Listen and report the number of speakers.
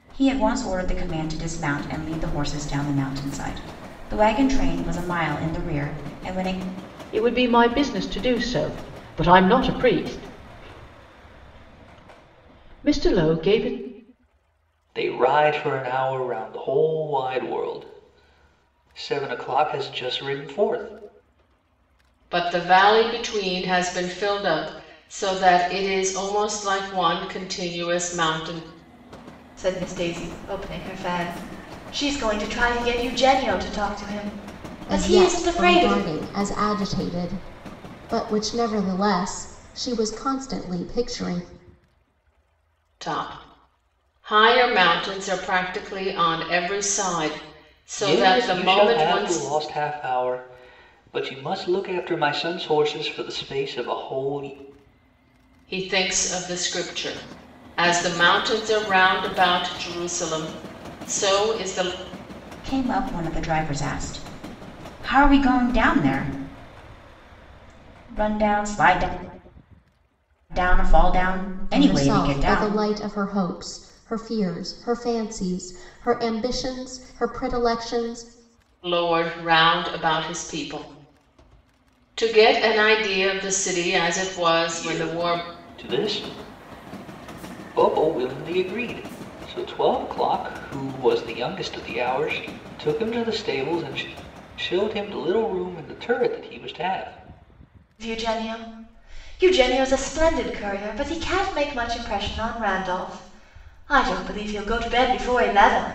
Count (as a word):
six